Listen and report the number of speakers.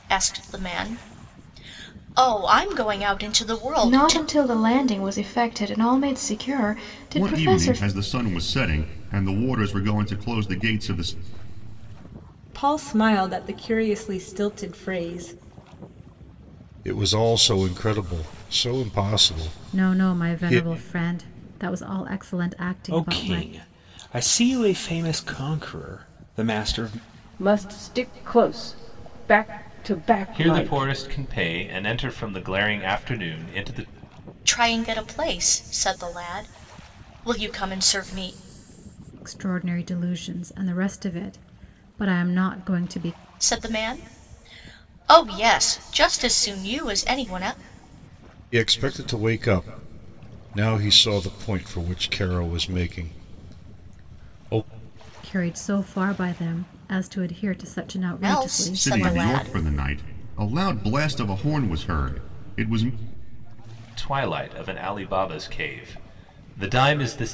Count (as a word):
nine